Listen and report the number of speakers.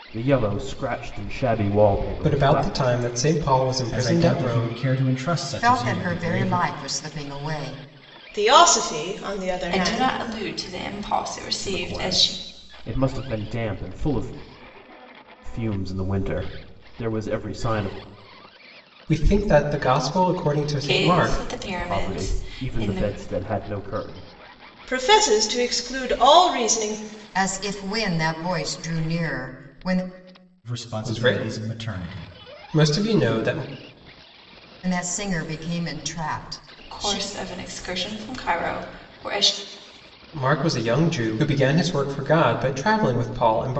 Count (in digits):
6